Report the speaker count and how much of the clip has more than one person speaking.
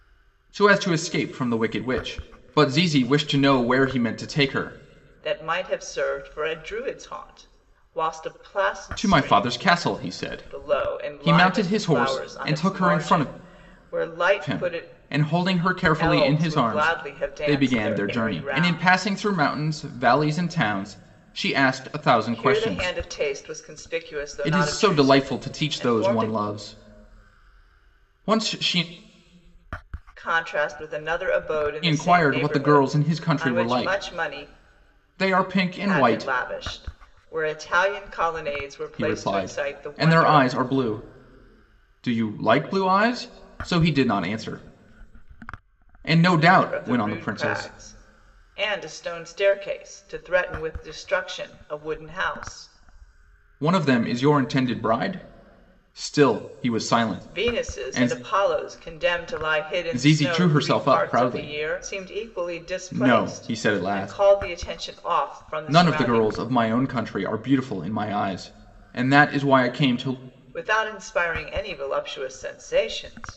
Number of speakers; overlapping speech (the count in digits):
2, about 29%